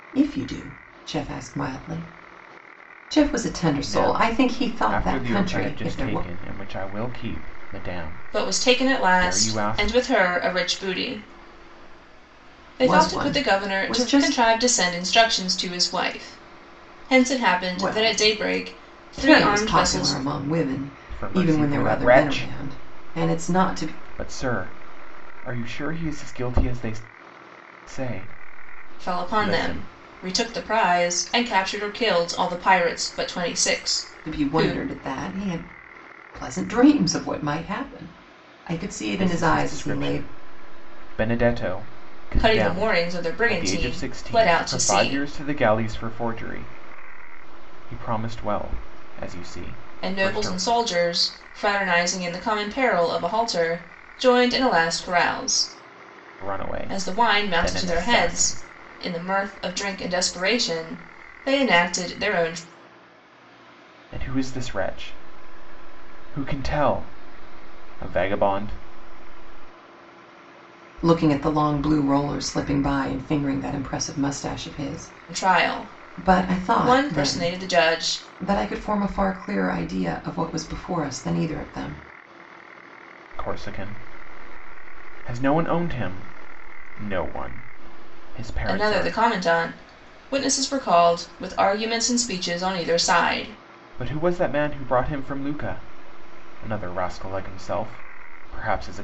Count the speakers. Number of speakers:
three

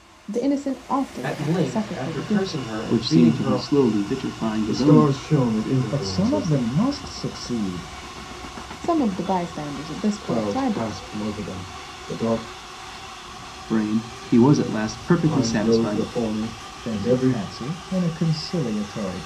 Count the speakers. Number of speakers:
five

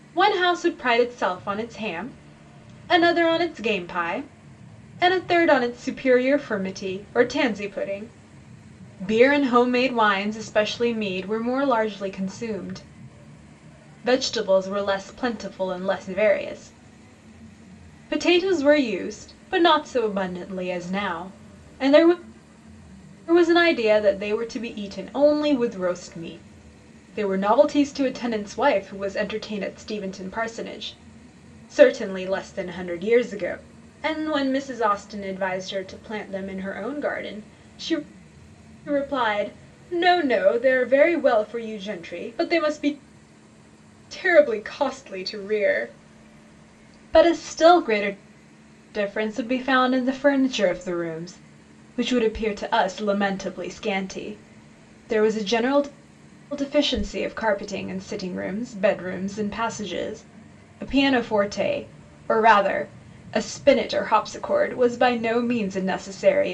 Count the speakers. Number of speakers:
one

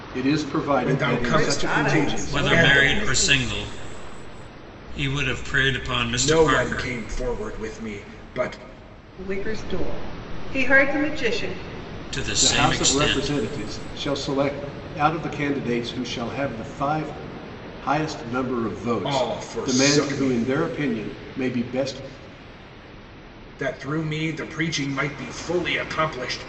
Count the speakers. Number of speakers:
four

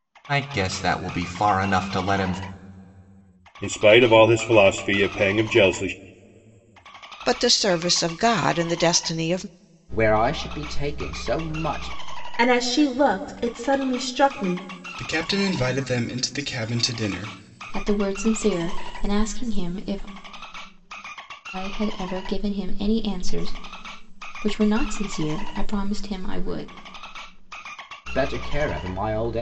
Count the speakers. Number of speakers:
seven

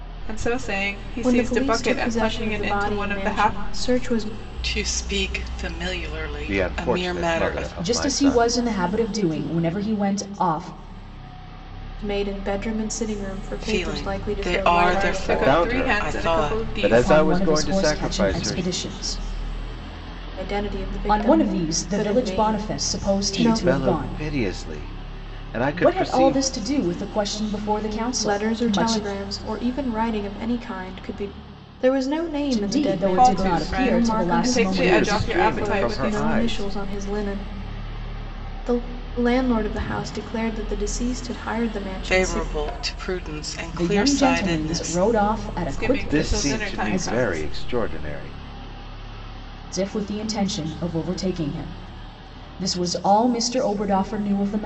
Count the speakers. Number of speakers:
five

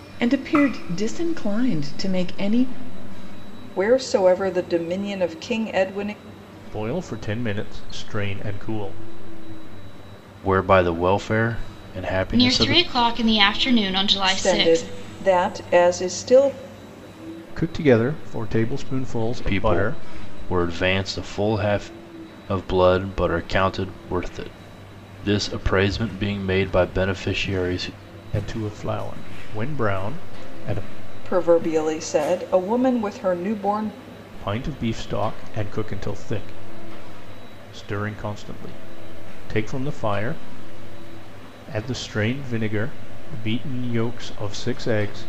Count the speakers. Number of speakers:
five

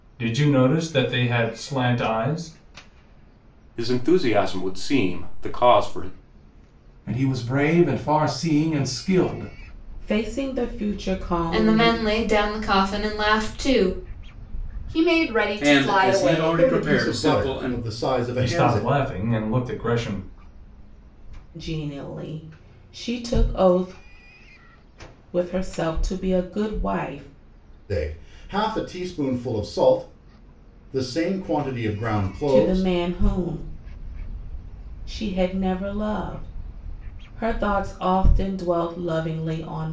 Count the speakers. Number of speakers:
eight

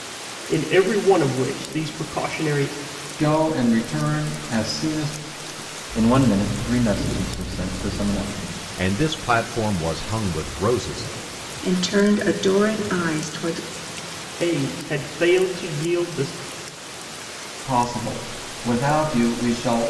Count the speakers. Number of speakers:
five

